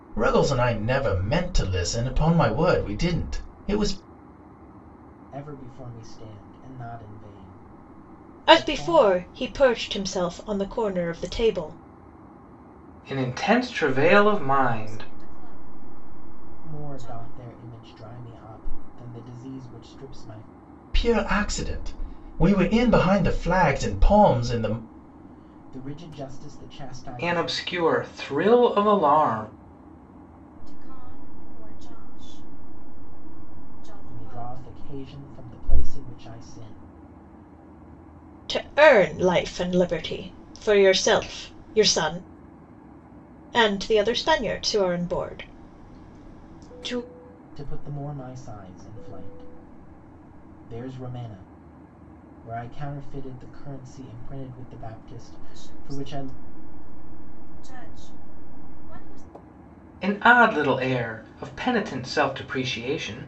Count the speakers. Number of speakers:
five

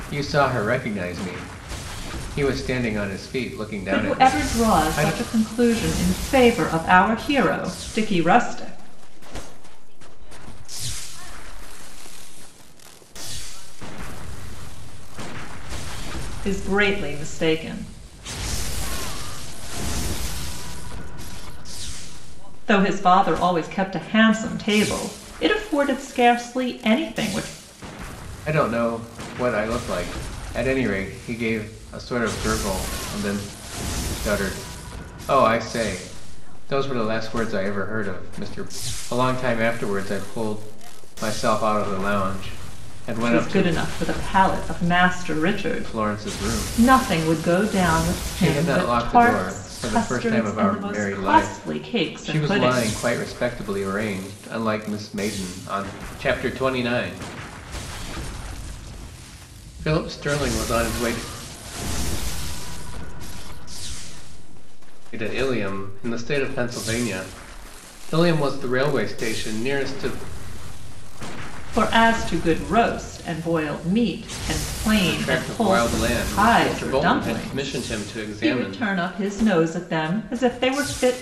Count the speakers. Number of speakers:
three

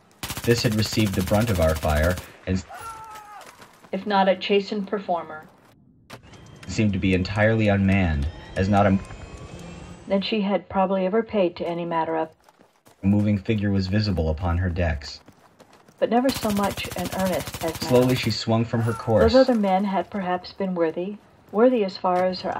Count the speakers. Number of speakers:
two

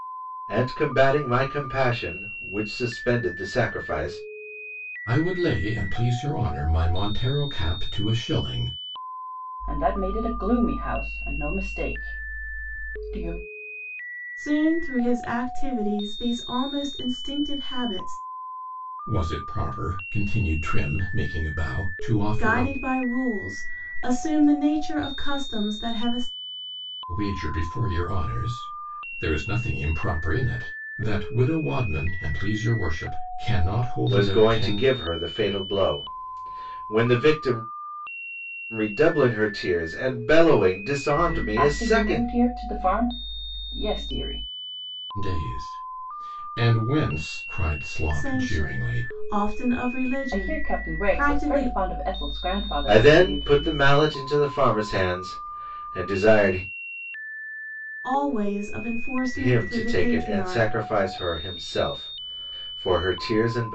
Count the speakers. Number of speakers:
four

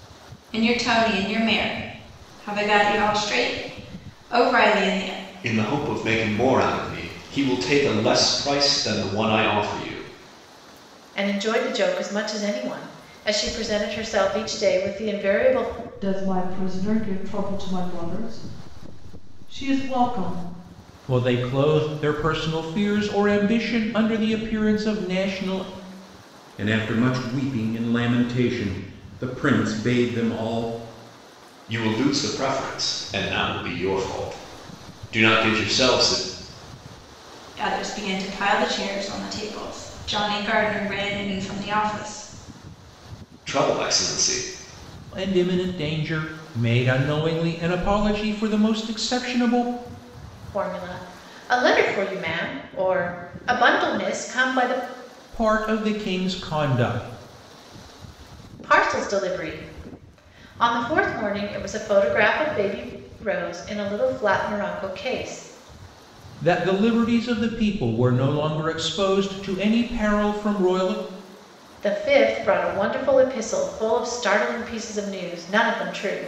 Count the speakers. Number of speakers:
six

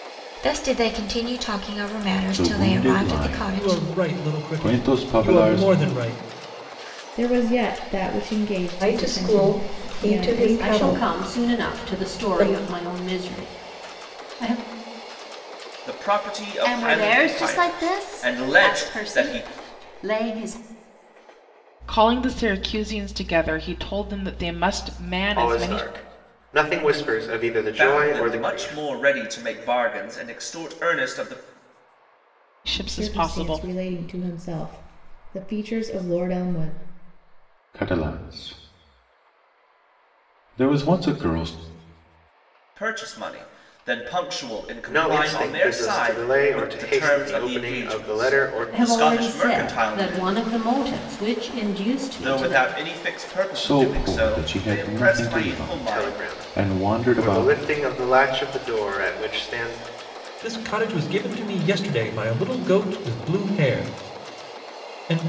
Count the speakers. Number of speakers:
ten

